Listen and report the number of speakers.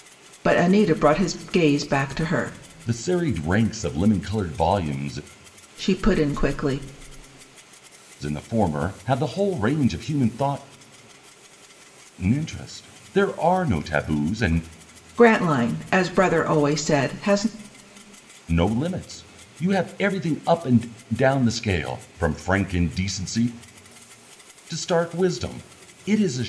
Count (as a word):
two